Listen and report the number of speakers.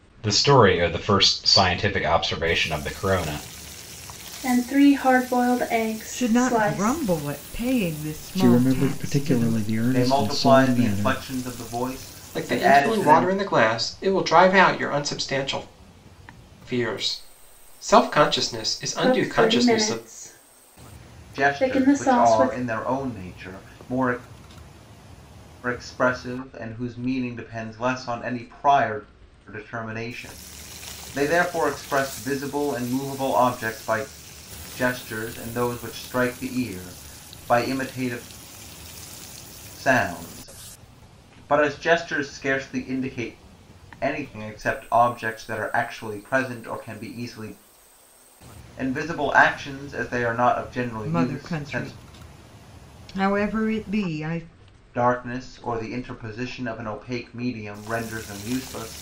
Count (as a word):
six